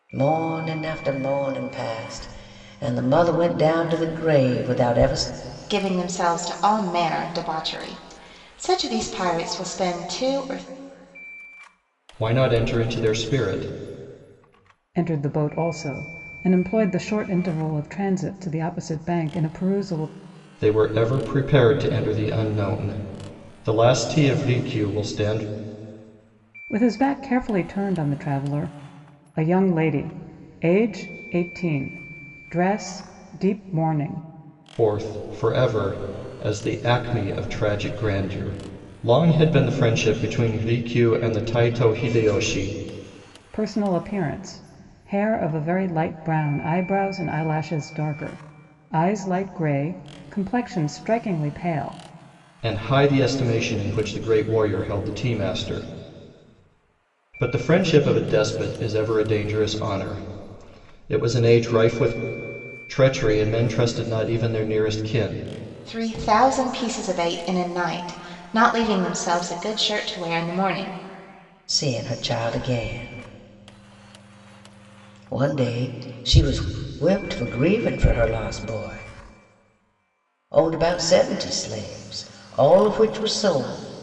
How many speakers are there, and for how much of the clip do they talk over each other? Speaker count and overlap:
four, no overlap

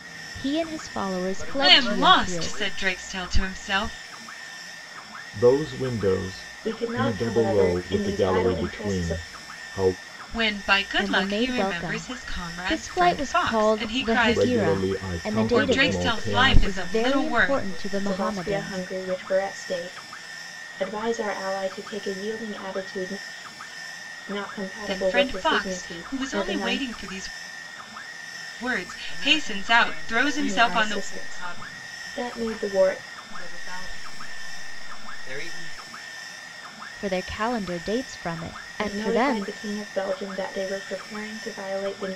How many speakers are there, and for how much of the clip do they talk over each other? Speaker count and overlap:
five, about 42%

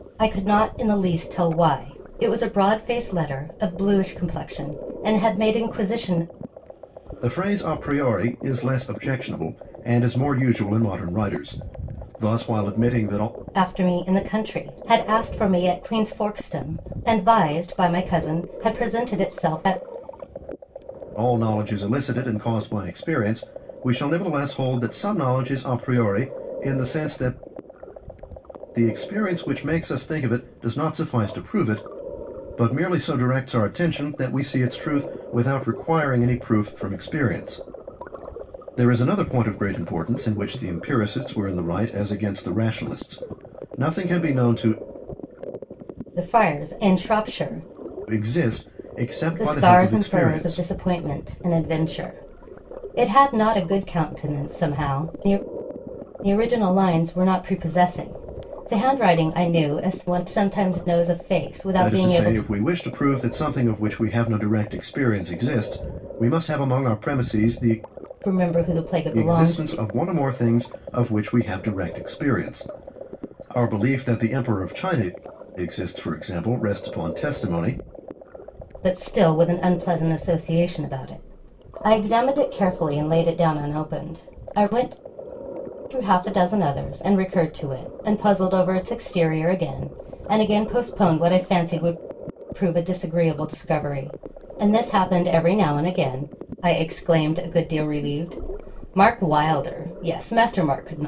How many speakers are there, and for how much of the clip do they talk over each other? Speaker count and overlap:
two, about 3%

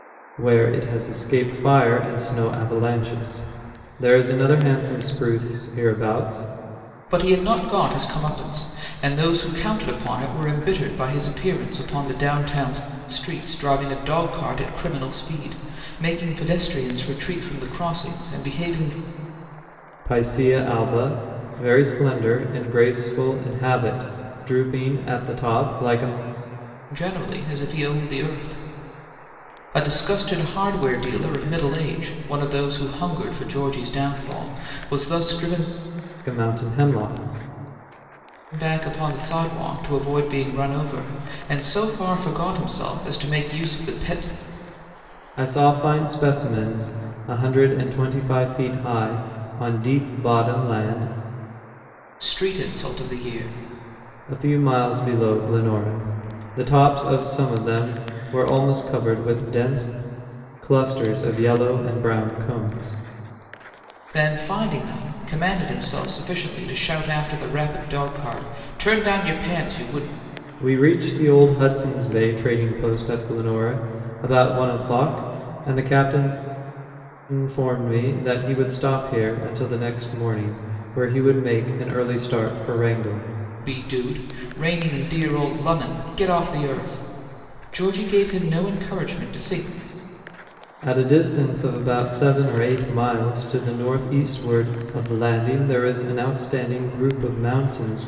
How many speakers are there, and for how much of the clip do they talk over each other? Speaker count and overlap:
two, no overlap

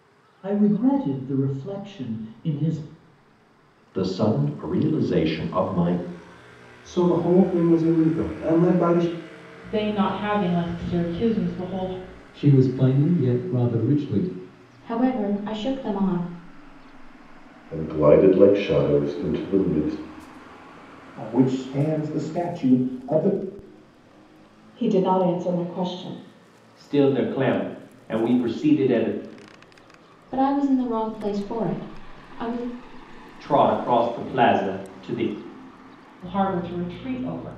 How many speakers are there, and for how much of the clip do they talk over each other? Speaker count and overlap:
ten, no overlap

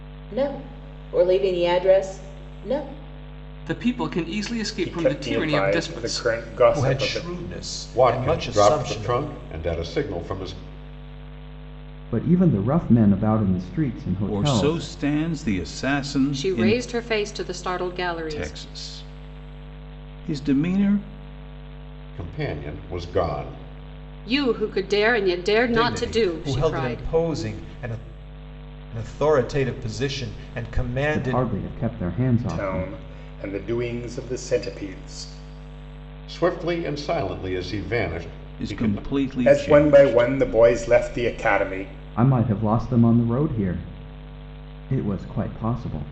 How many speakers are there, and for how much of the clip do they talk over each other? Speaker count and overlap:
eight, about 19%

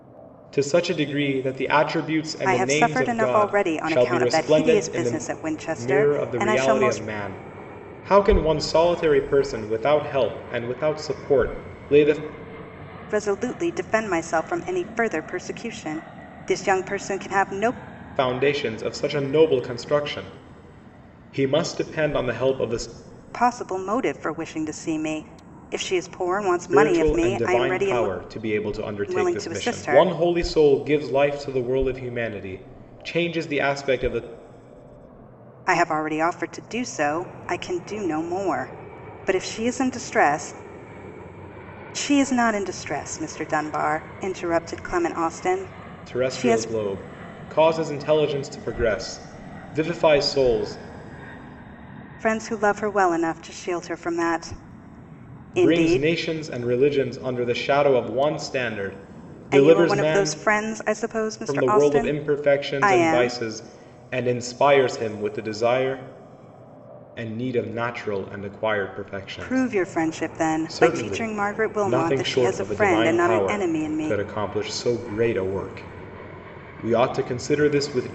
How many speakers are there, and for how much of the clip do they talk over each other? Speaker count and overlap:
two, about 19%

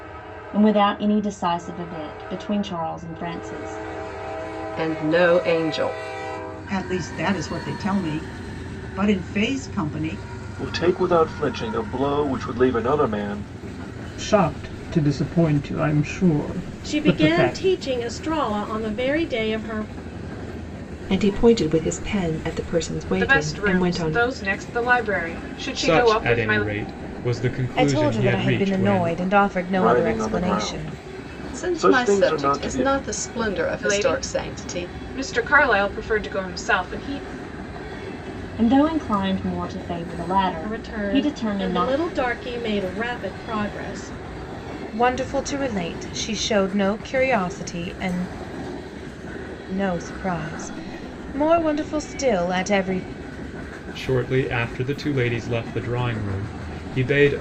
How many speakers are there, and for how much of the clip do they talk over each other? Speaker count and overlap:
ten, about 16%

